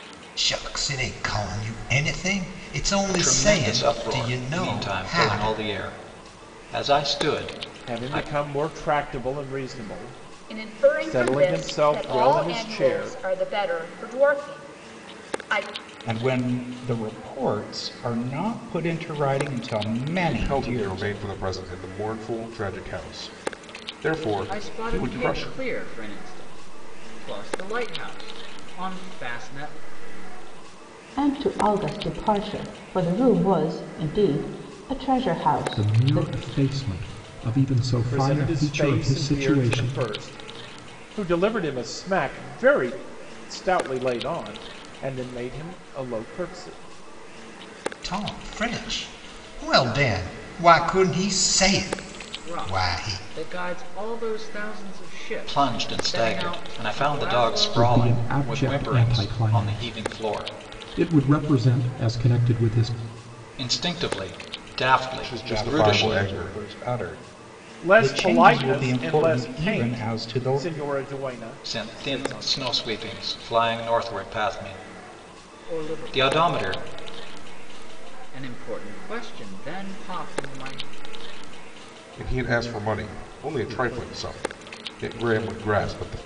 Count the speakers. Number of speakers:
9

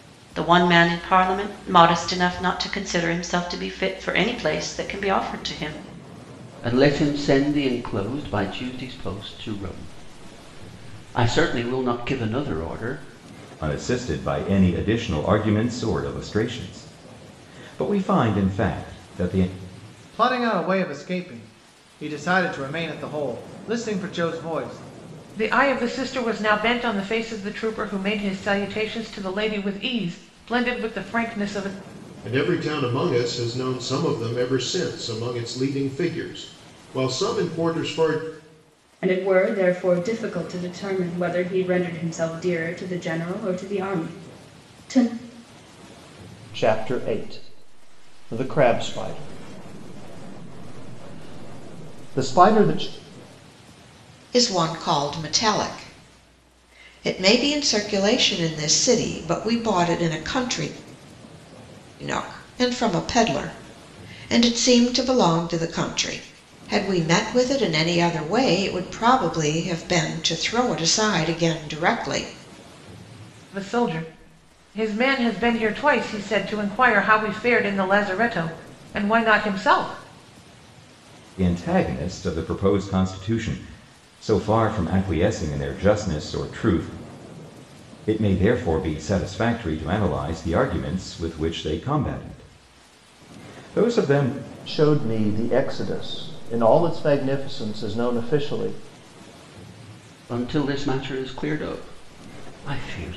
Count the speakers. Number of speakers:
9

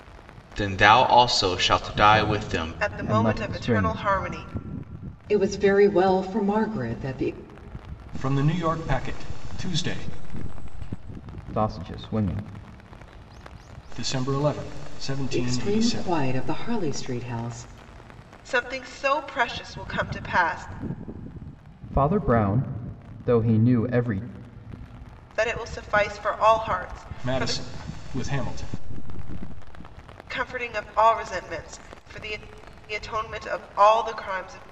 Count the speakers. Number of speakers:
5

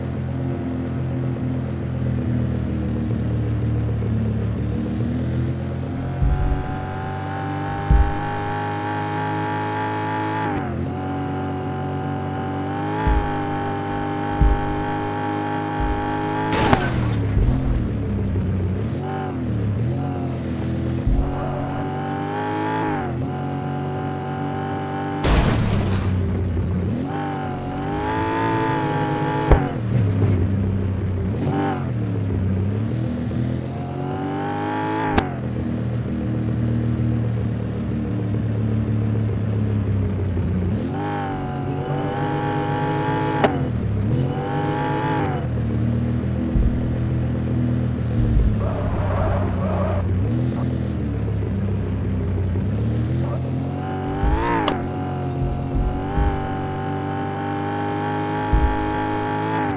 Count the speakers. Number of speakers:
0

